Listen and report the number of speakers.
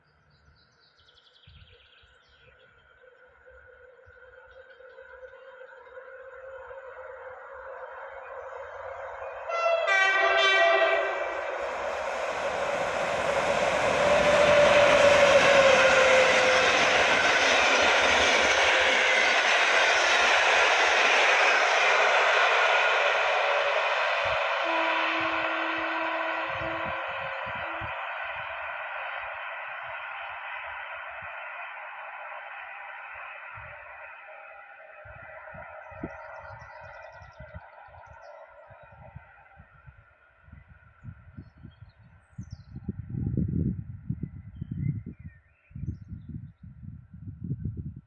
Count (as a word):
zero